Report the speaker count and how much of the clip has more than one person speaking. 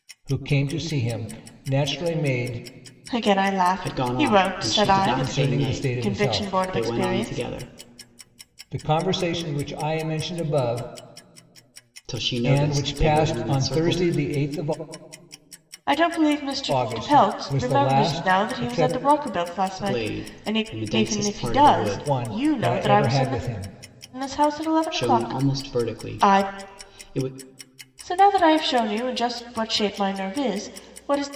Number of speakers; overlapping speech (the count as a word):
three, about 40%